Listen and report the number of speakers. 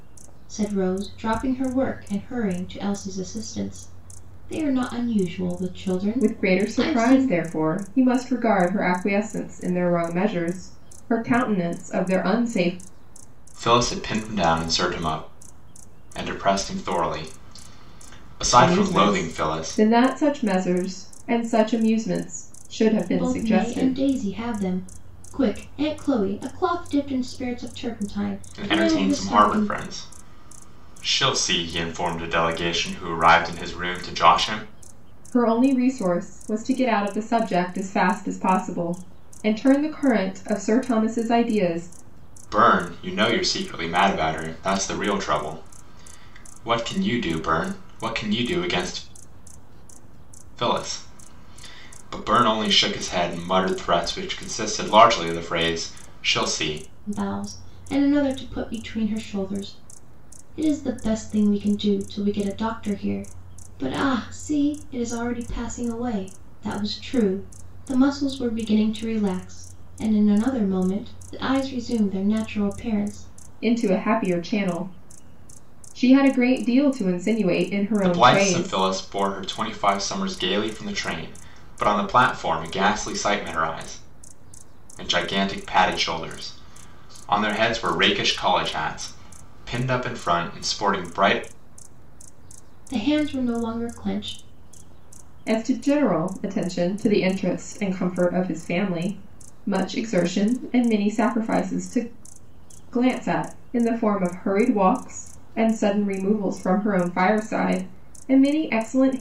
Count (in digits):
3